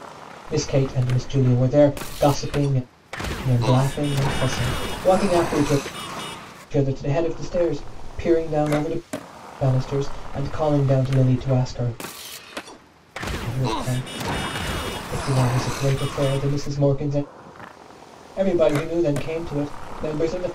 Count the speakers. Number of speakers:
1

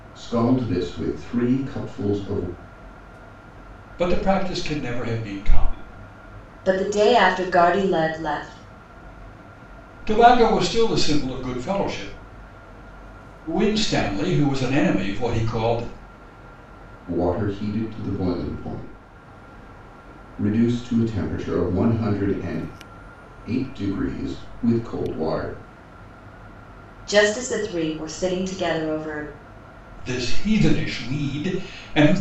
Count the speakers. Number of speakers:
3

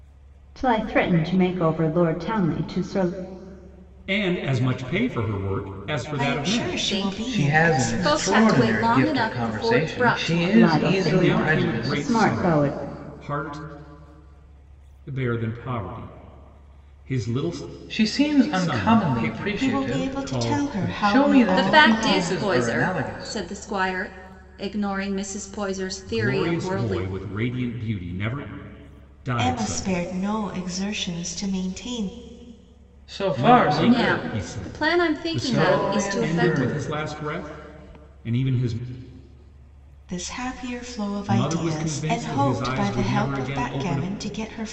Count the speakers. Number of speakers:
5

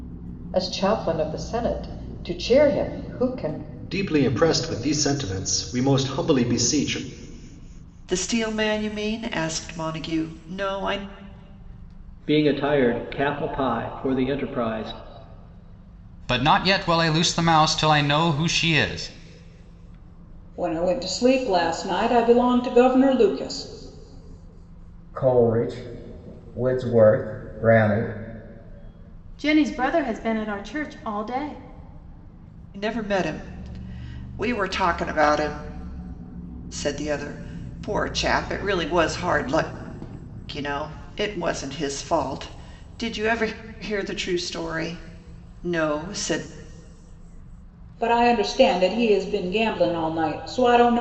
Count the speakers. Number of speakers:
8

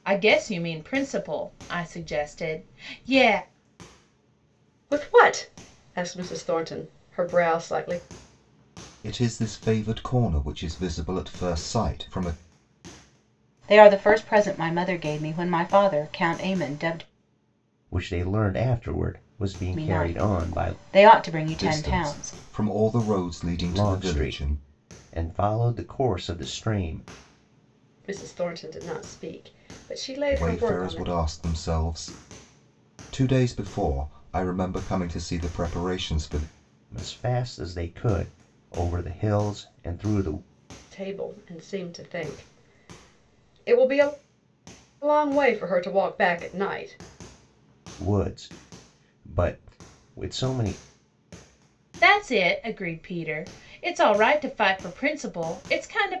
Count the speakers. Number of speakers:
5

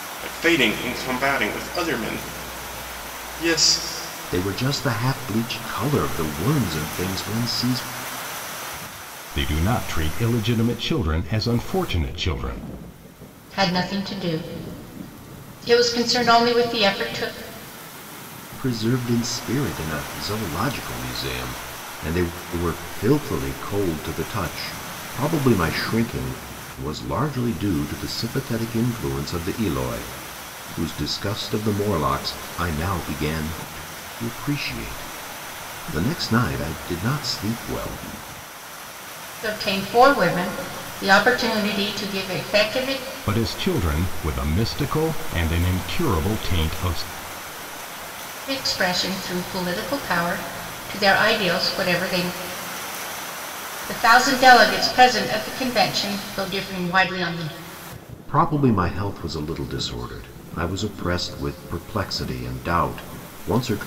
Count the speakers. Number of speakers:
4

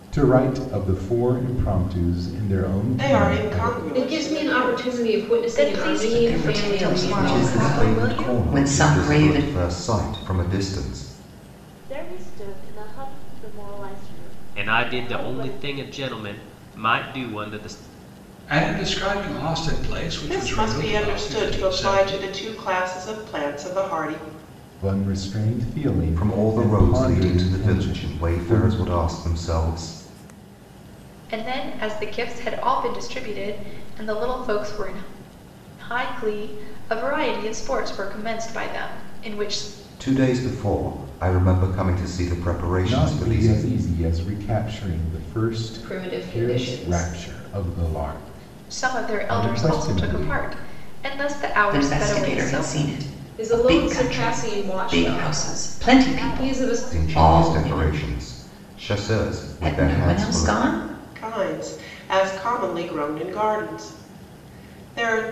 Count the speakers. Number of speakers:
9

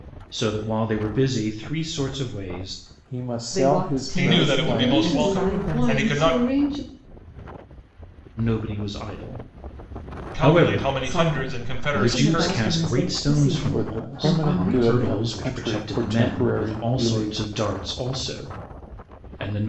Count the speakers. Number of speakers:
5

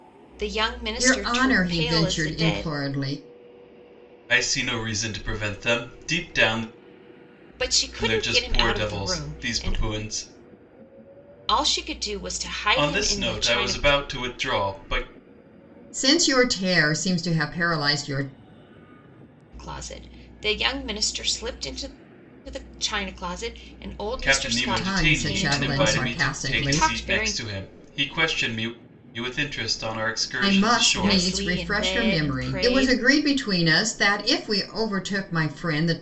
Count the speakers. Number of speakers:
3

